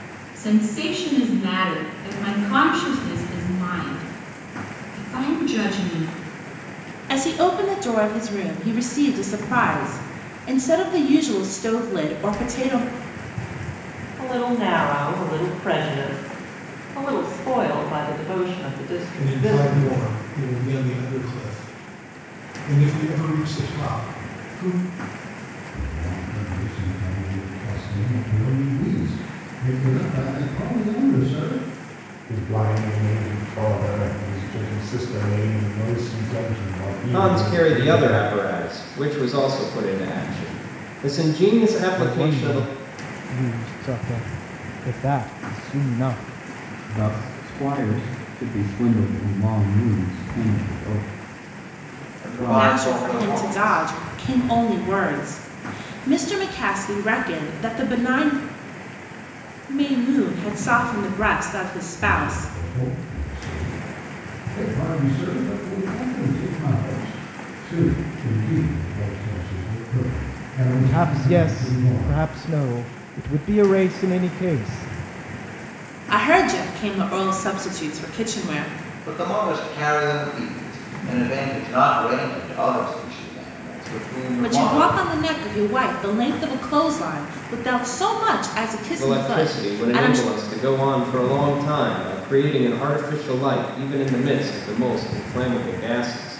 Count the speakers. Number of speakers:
10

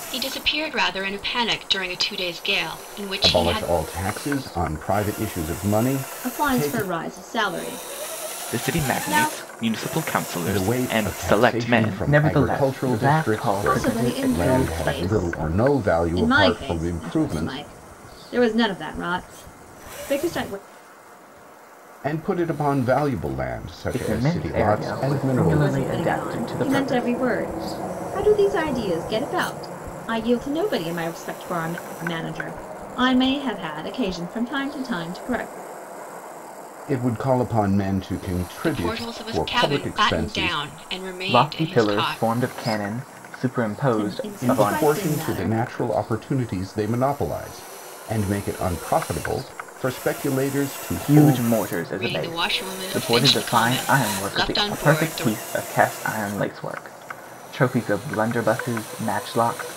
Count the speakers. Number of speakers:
4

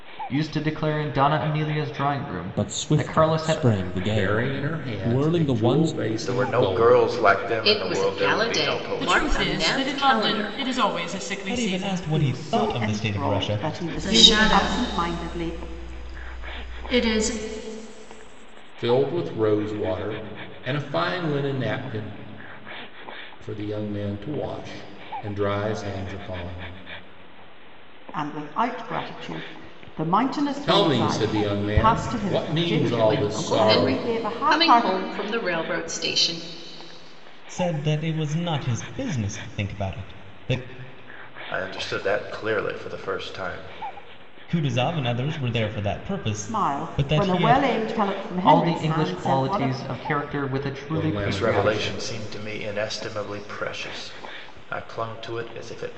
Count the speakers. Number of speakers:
9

